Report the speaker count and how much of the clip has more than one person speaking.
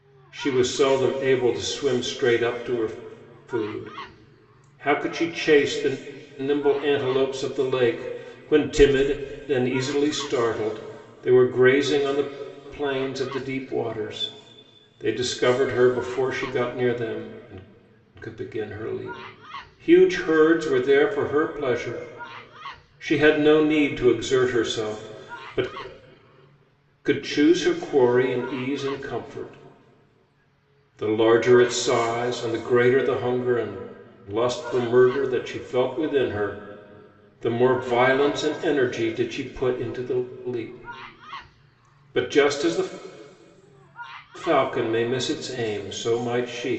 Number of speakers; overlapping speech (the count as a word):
one, no overlap